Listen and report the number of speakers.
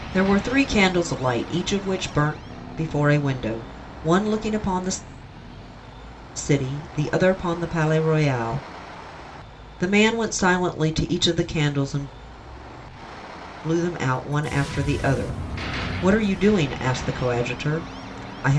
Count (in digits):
1